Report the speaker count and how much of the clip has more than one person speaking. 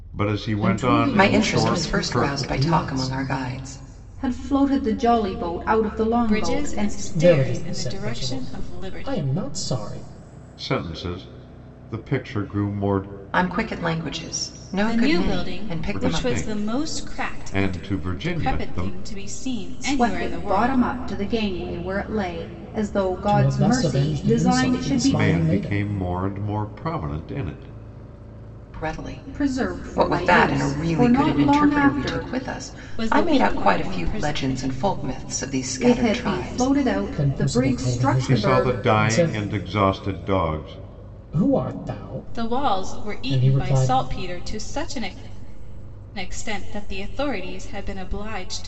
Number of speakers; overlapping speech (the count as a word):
five, about 46%